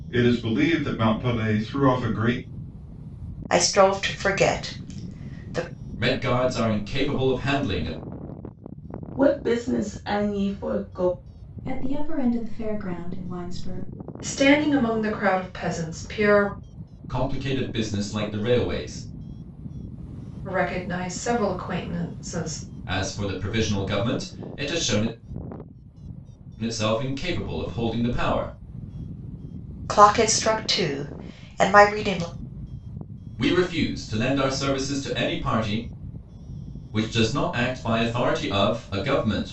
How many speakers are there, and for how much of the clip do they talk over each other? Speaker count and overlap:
6, no overlap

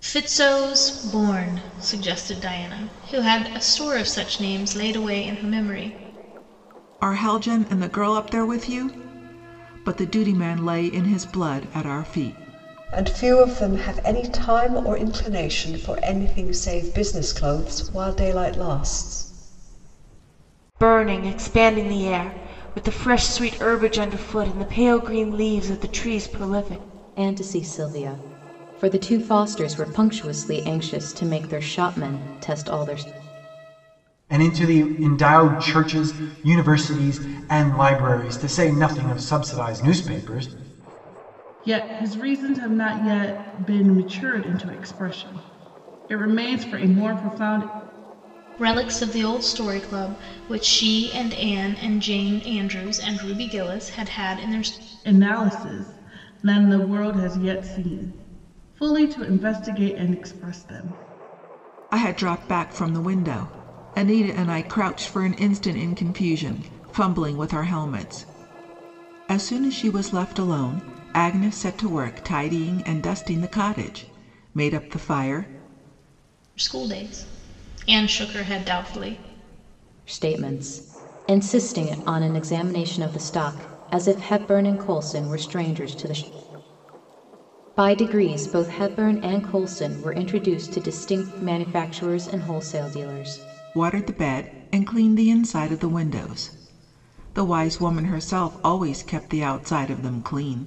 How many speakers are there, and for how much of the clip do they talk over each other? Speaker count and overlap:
7, no overlap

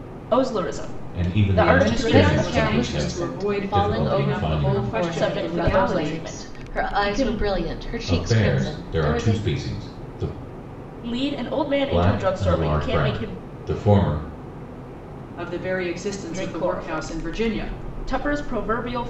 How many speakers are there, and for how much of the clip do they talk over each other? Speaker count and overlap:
4, about 56%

